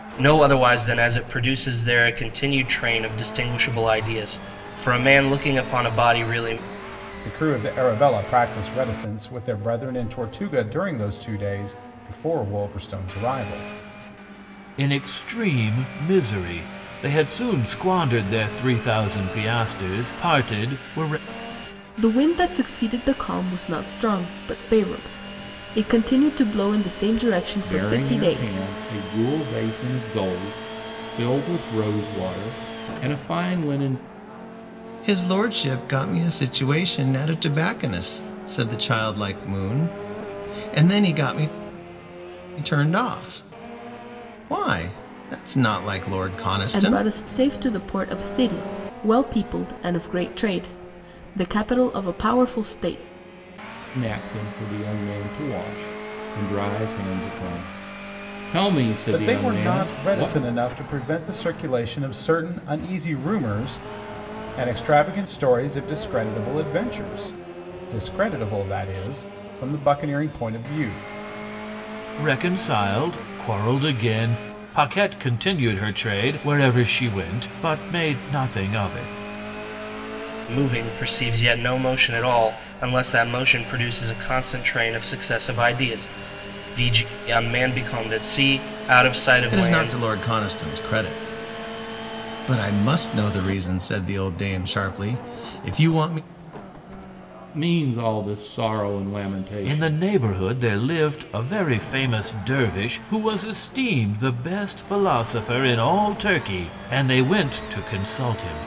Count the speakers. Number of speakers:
6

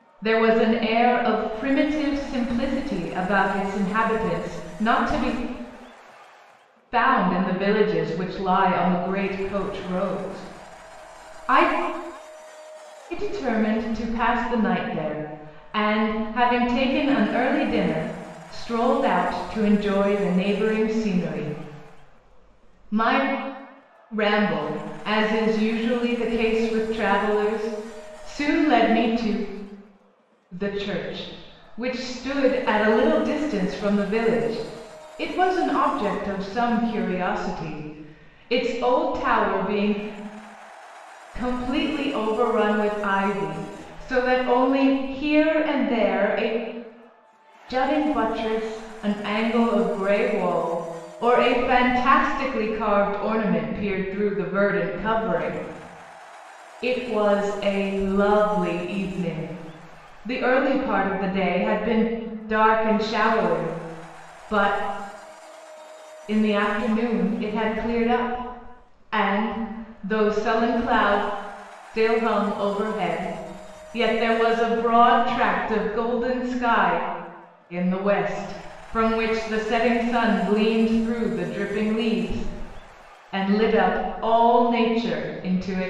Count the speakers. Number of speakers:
1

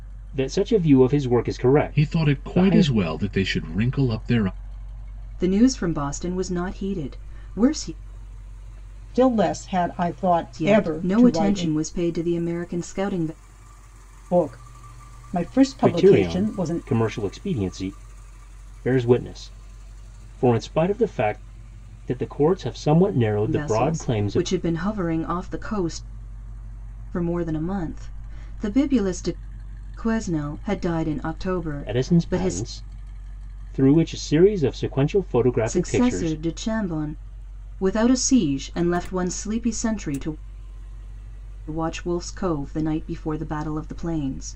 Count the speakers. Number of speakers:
4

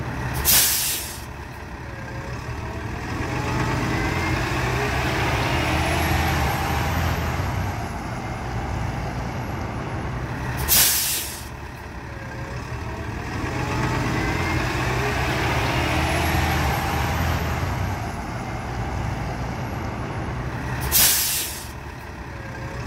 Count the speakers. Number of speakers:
0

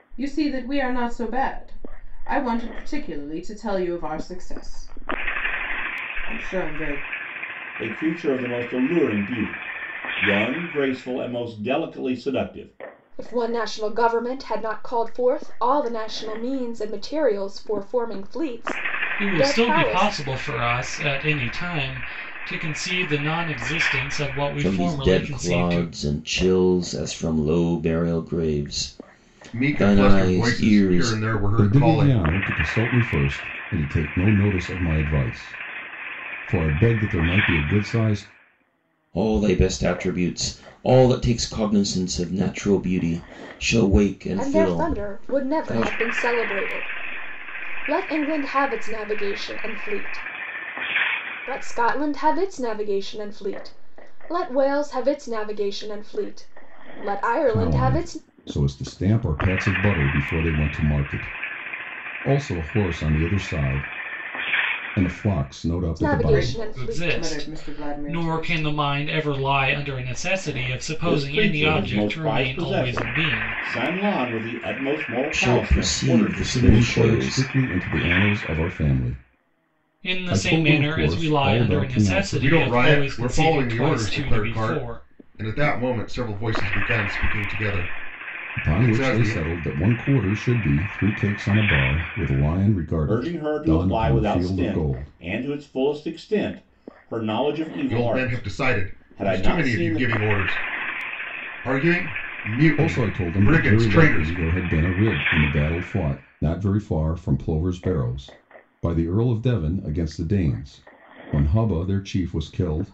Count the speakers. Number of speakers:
7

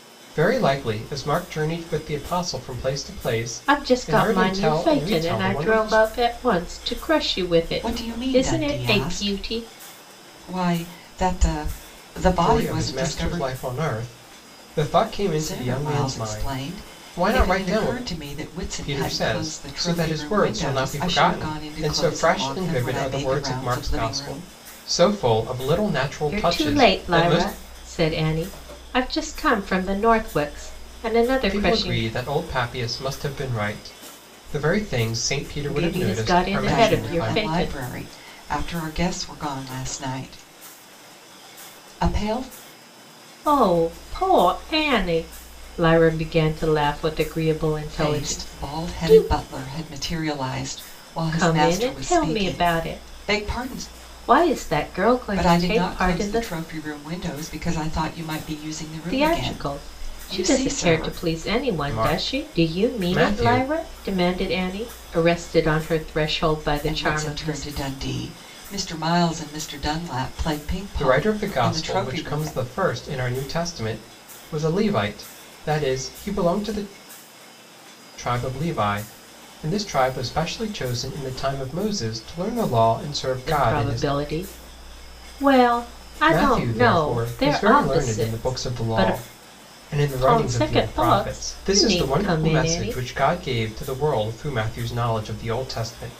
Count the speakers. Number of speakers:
3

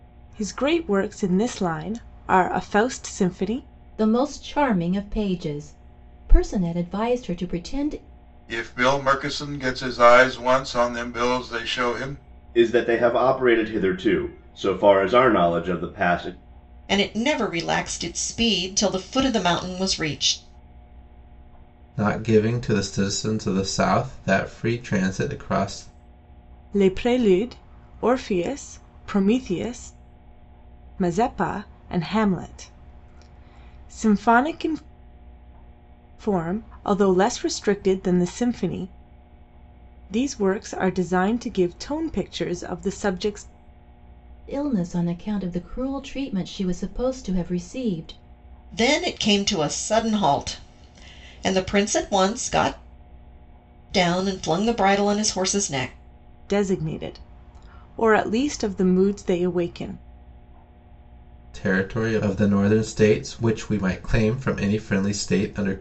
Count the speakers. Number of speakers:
6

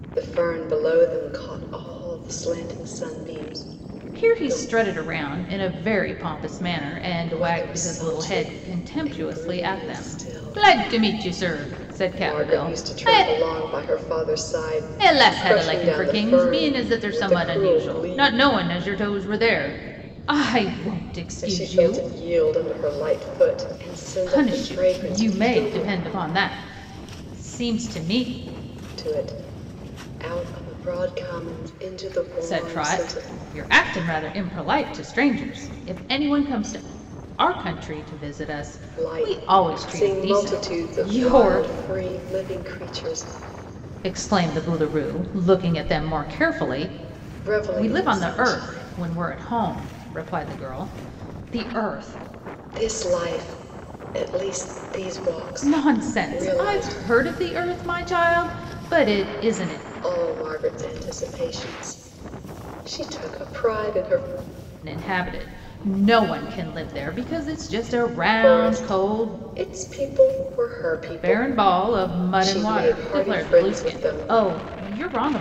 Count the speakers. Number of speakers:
2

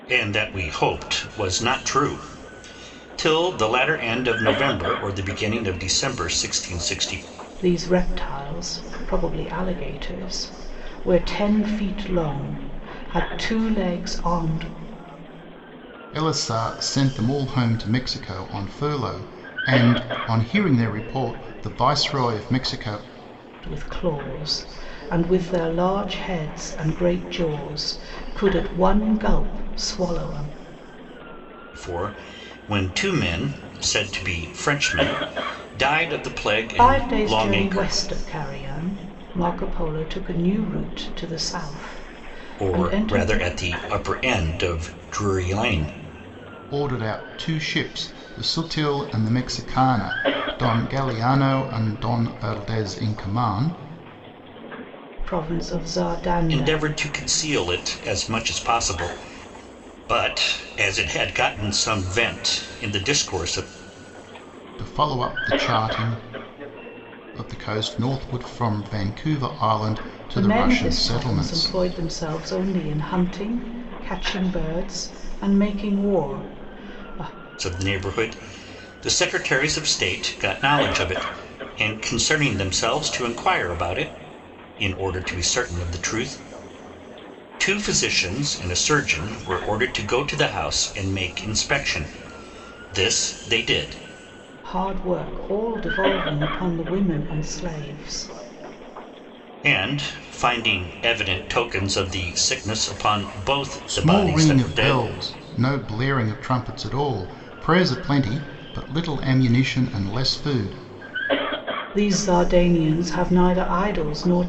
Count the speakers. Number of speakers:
3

